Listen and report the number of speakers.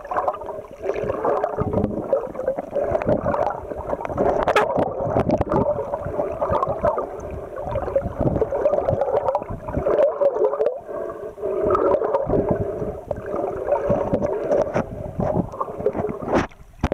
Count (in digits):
0